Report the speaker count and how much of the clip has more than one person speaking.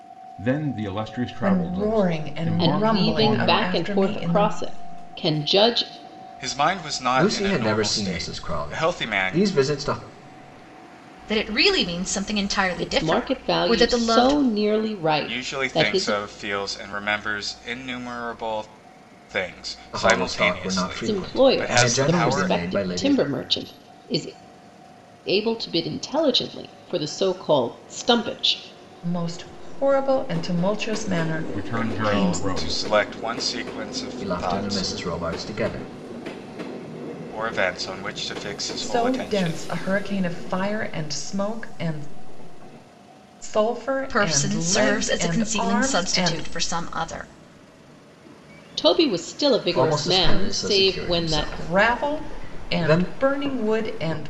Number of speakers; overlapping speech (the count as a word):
six, about 37%